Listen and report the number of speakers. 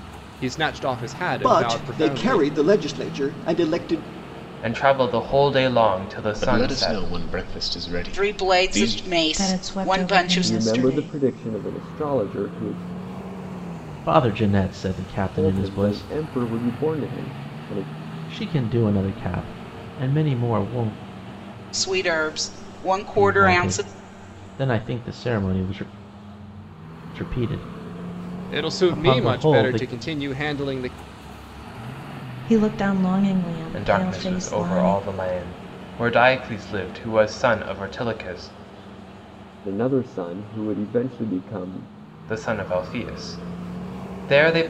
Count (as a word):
eight